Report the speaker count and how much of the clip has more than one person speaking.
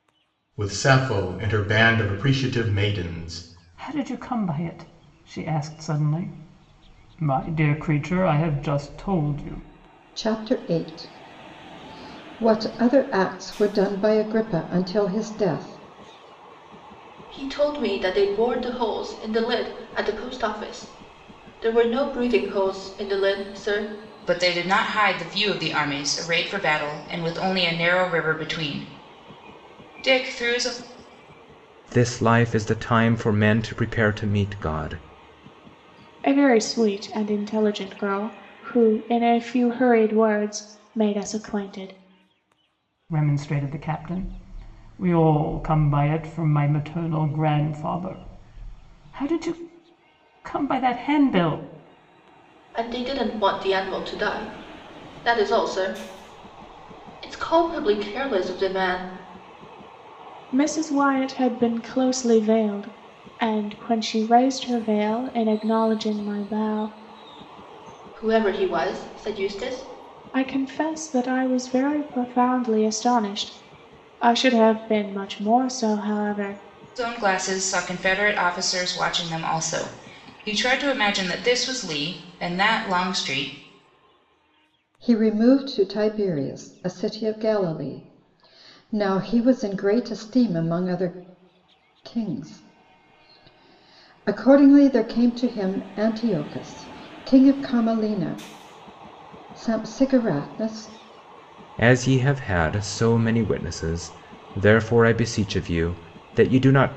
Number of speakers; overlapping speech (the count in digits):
7, no overlap